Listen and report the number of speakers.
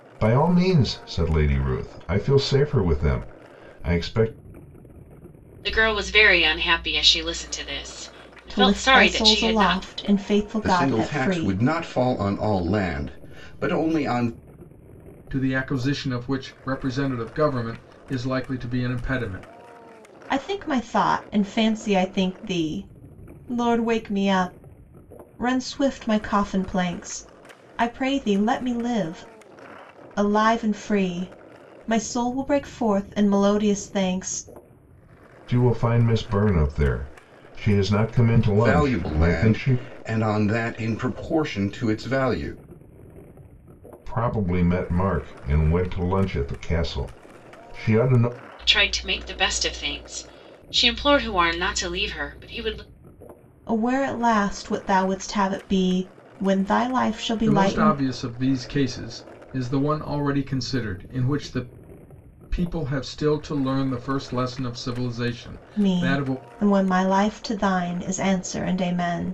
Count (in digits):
5